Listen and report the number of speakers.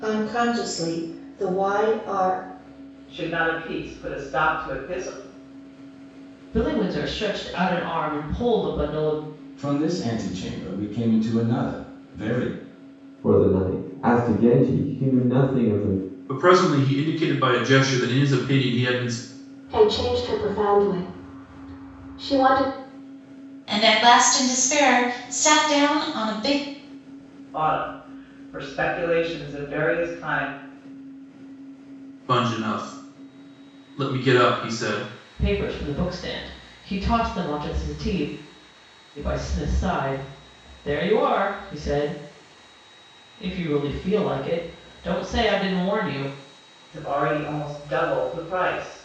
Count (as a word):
eight